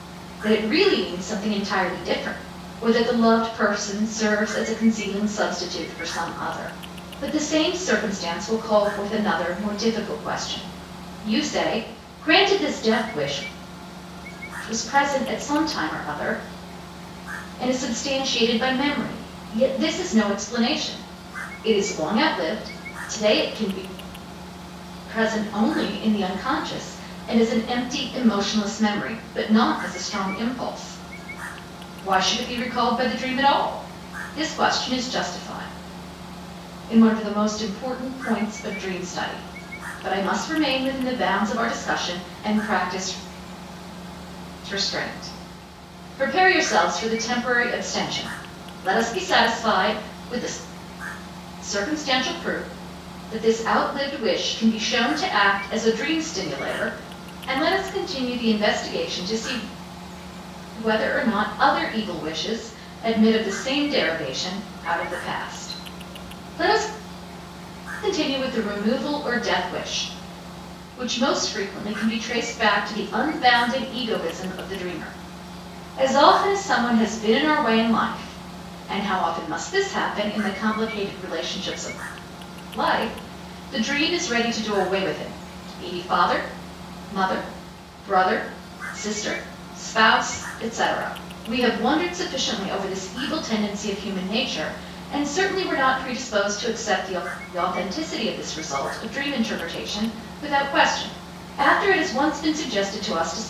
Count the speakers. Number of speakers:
1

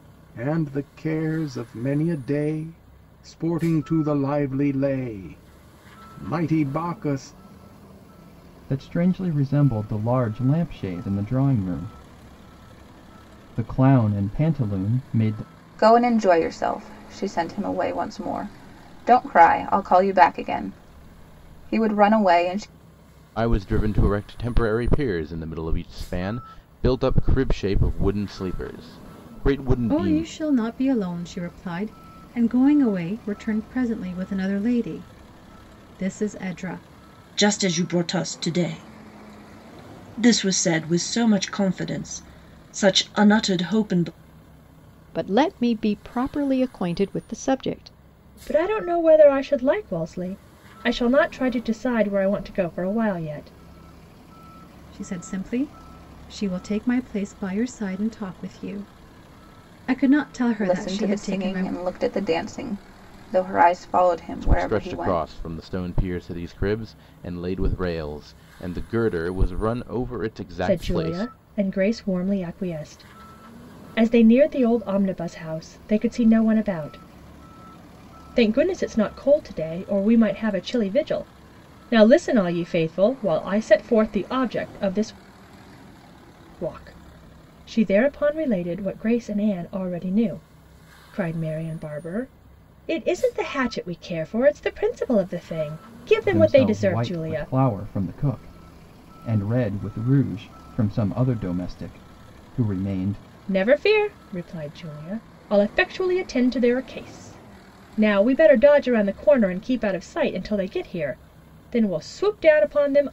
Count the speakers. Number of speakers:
8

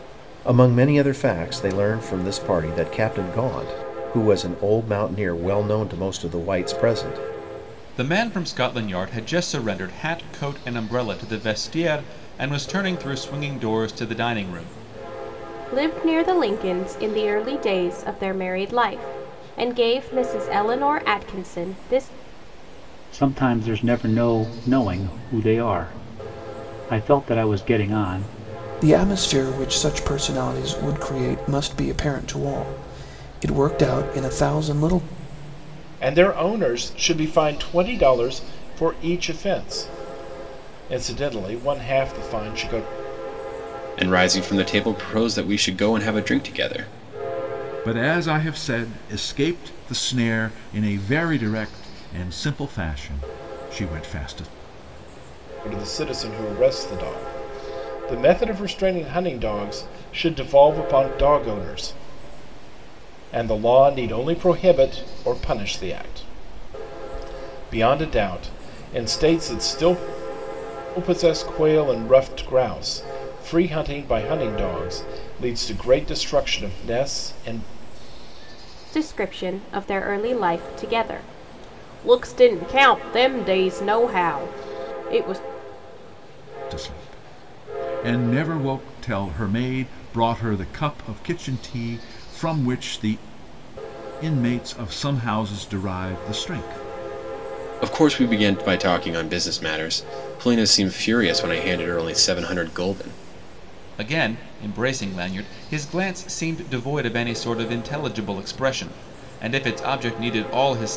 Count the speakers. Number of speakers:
8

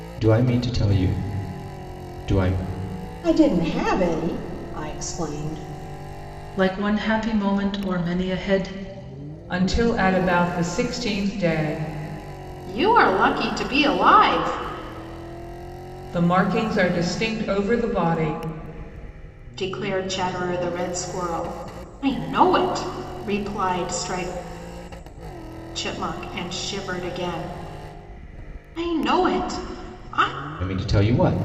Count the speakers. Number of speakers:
5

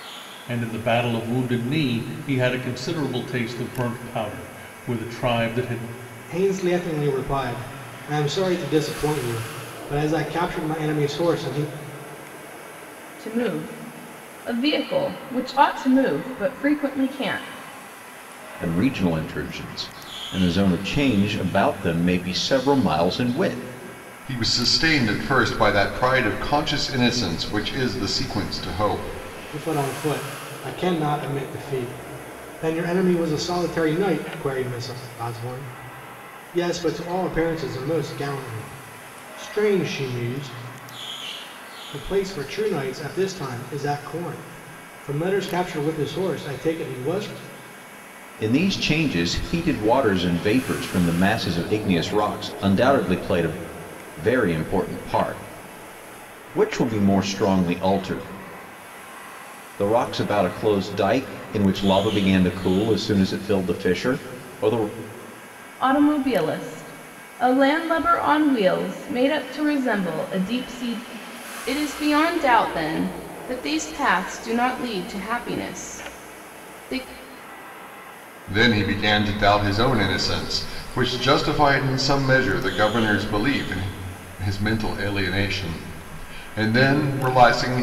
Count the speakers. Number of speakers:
5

